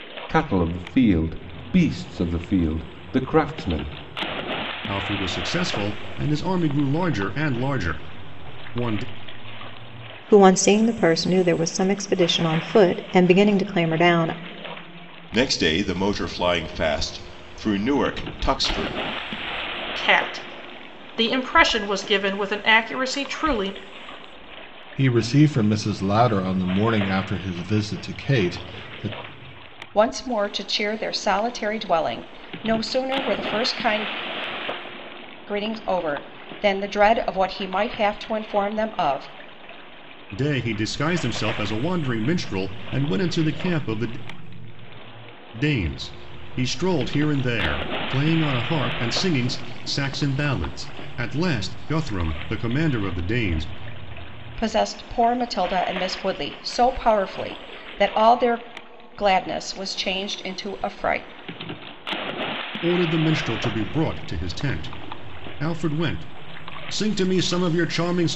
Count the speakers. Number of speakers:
seven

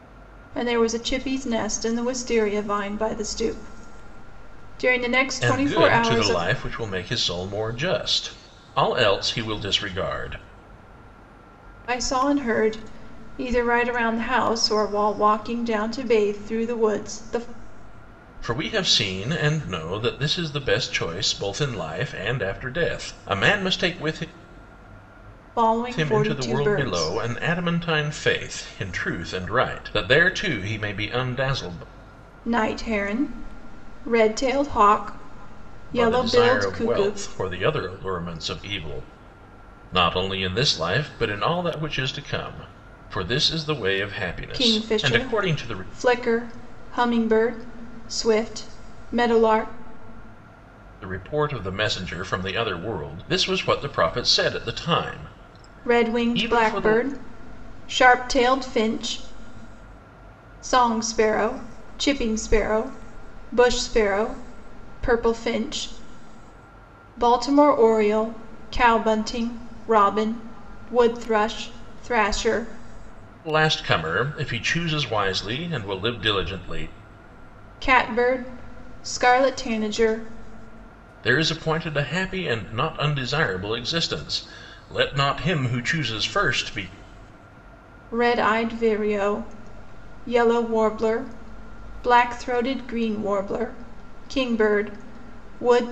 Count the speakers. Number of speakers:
two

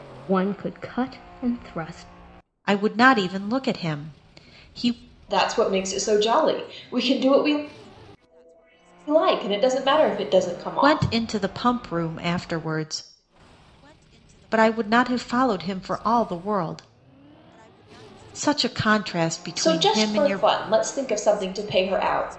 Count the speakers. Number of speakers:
three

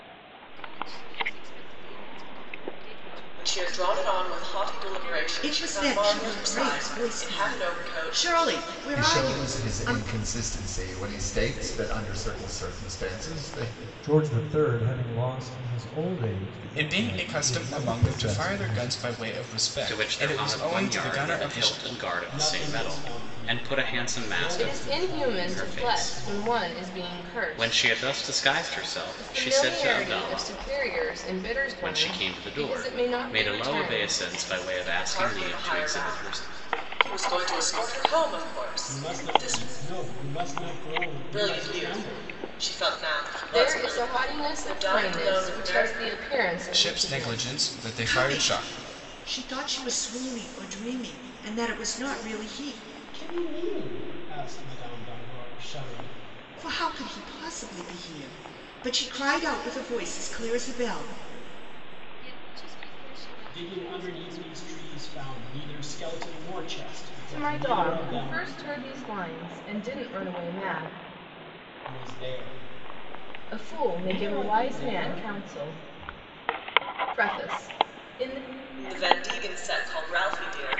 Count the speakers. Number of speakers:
nine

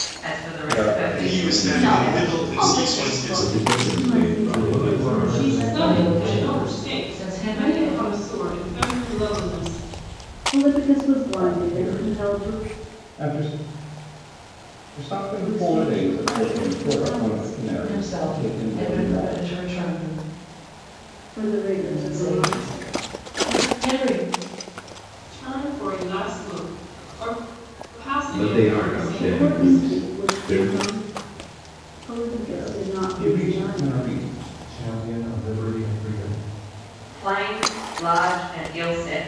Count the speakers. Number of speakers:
nine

